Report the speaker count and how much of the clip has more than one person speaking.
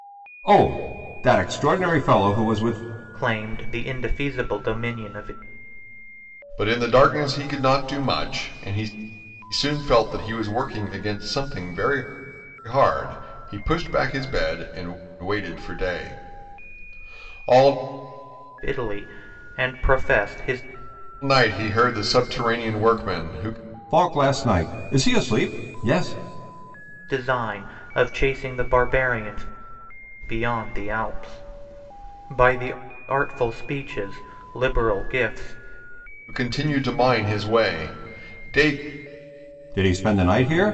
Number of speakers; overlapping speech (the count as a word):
three, no overlap